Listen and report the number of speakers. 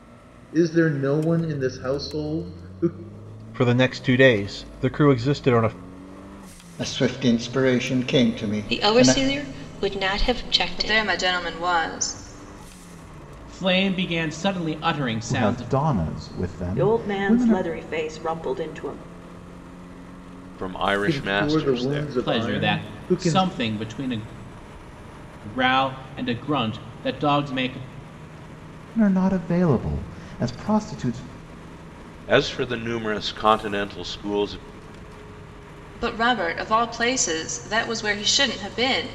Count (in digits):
9